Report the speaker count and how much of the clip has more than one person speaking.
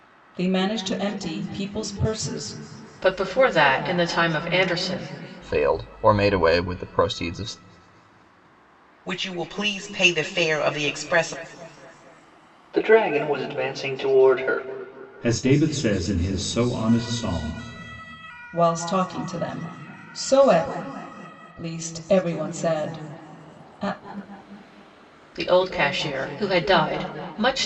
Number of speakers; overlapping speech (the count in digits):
6, no overlap